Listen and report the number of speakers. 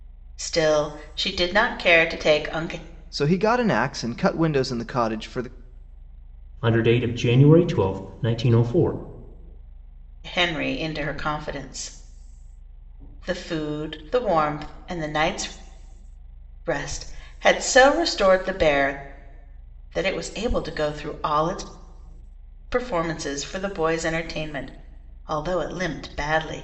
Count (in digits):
3